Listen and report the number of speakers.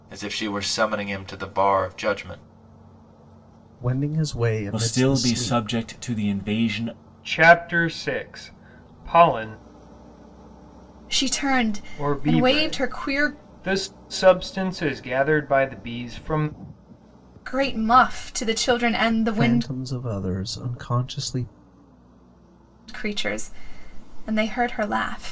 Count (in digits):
5